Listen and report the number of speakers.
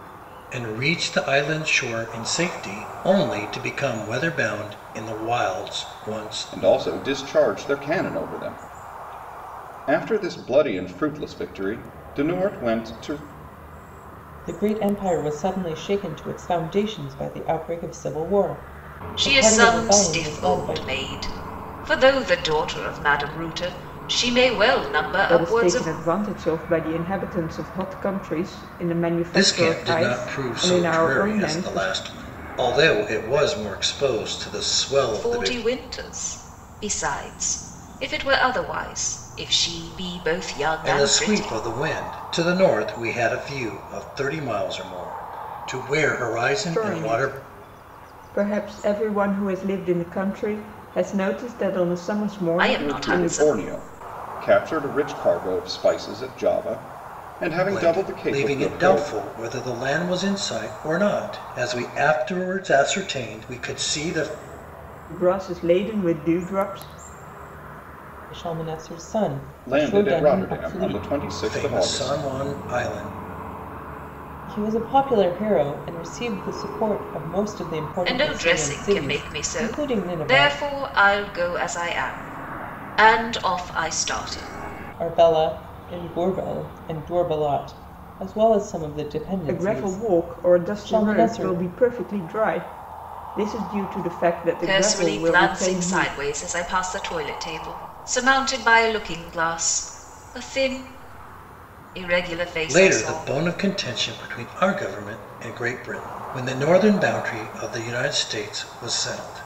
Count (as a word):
five